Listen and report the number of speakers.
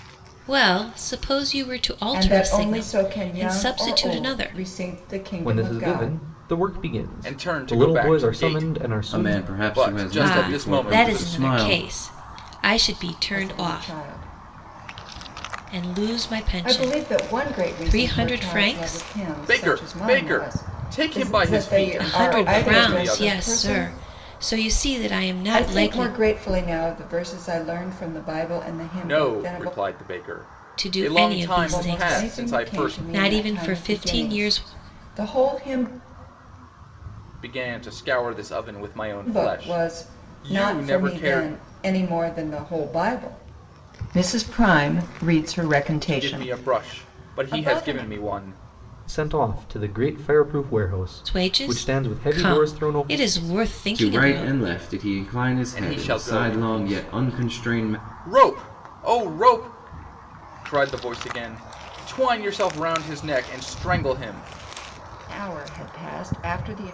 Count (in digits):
5